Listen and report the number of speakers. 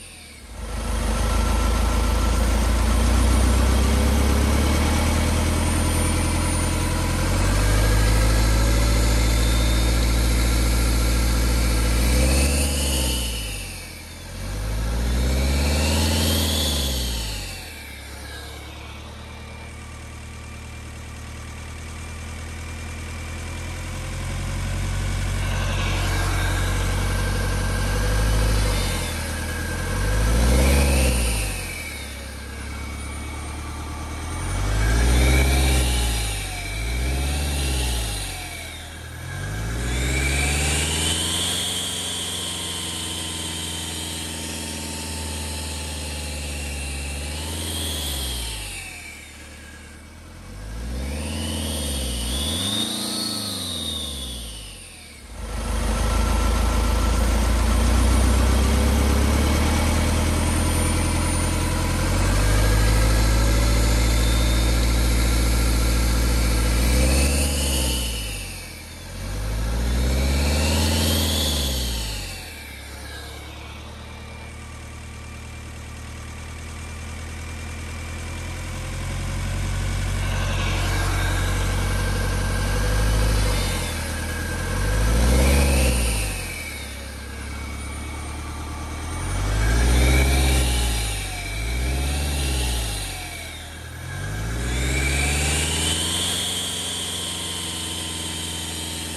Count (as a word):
zero